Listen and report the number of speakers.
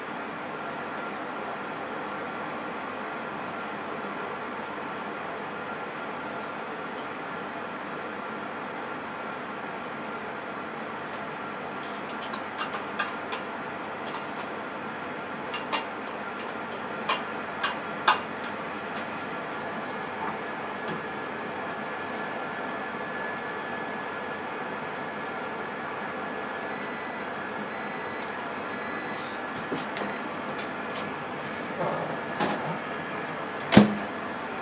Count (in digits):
0